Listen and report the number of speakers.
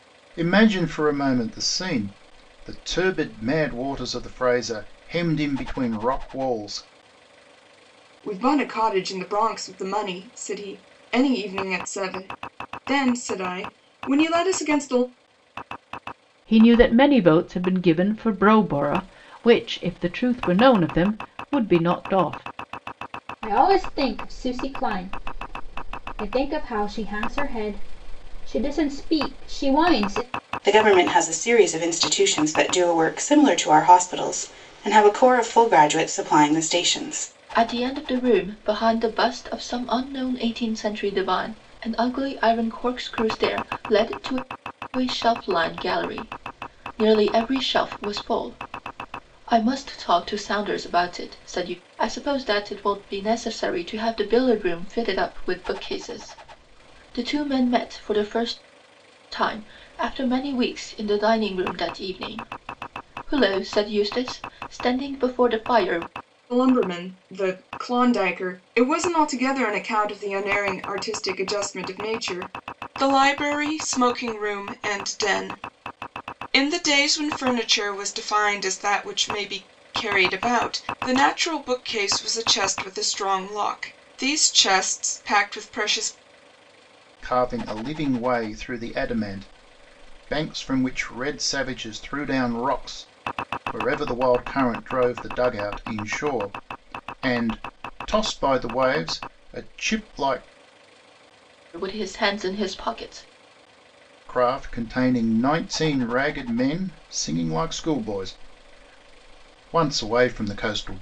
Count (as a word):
six